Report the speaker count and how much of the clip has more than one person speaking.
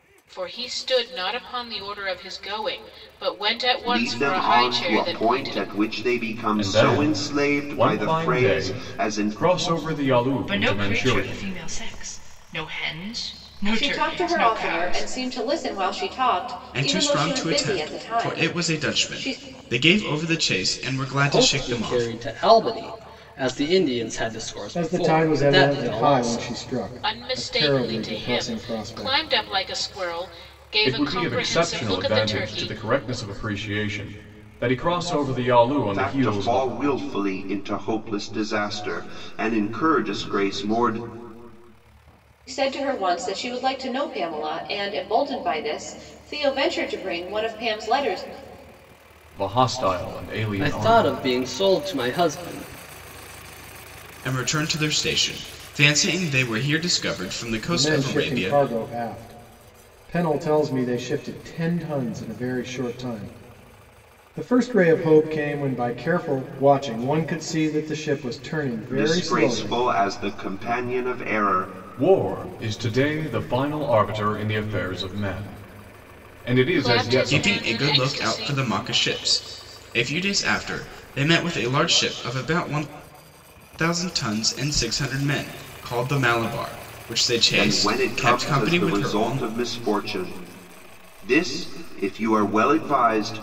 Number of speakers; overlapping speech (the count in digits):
8, about 25%